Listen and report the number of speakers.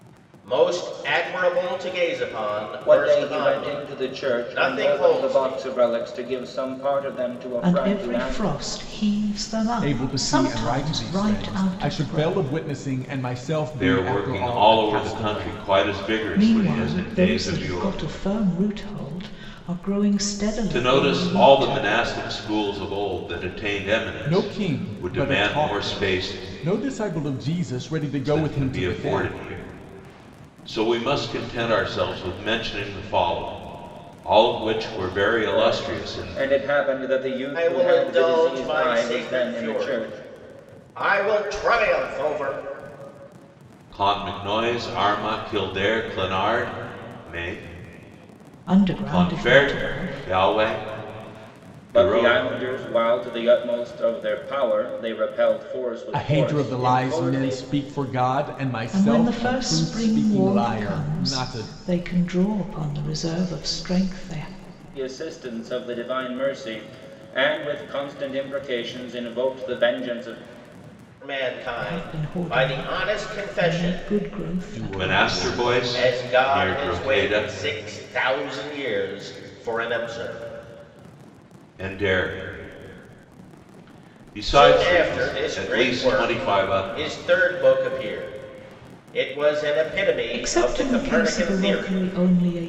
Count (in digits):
5